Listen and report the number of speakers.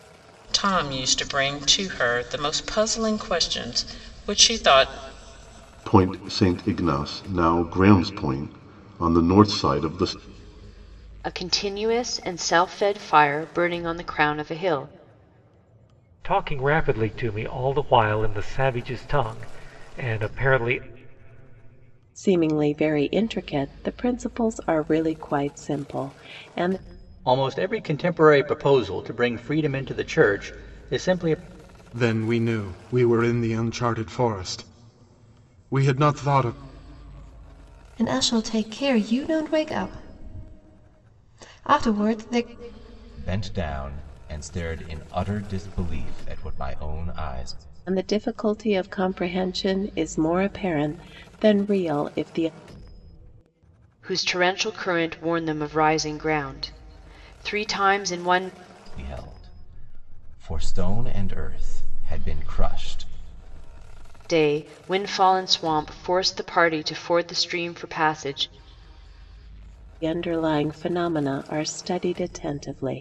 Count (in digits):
9